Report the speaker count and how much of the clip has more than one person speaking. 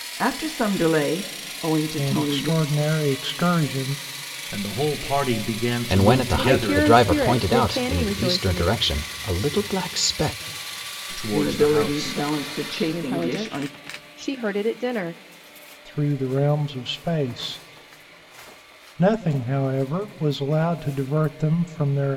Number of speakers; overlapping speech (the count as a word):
five, about 23%